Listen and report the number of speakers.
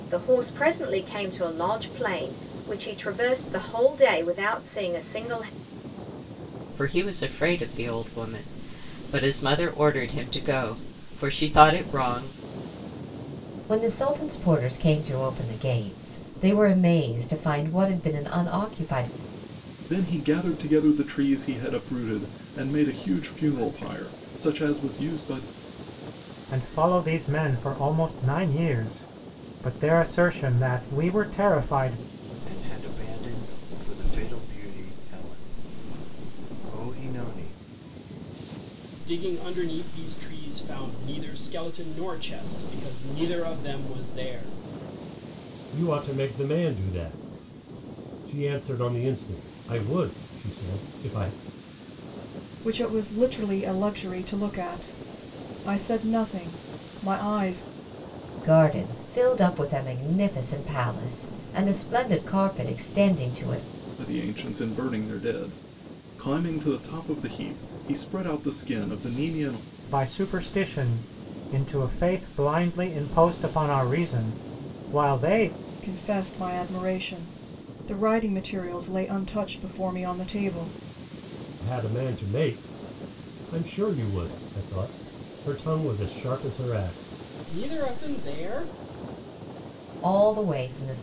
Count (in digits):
9